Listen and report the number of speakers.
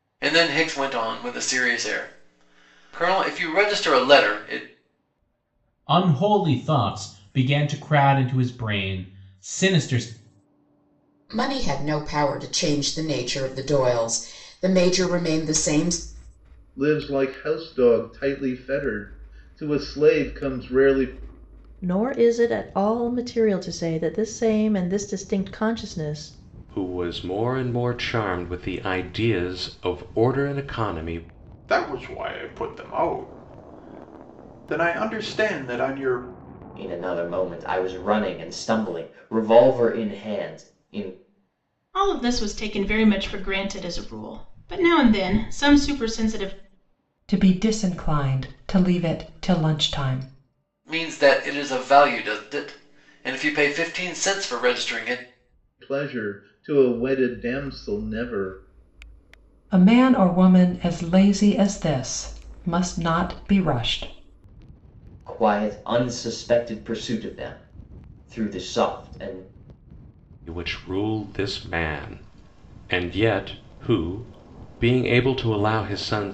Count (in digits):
10